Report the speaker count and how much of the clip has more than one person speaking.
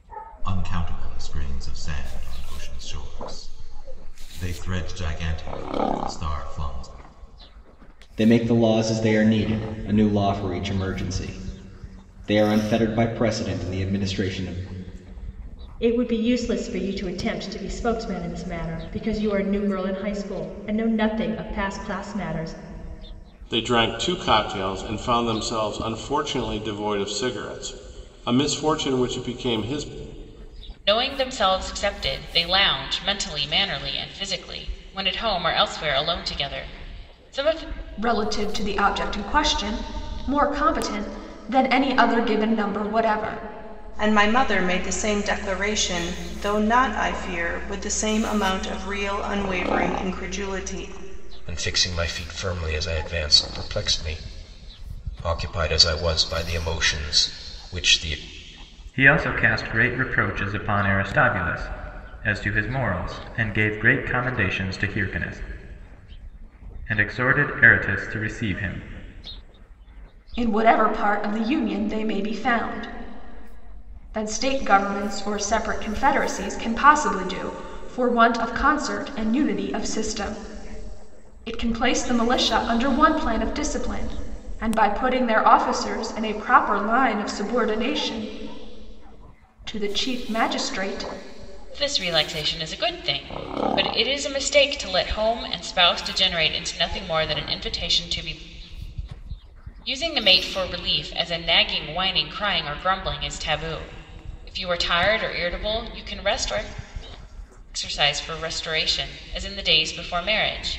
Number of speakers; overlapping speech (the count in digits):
9, no overlap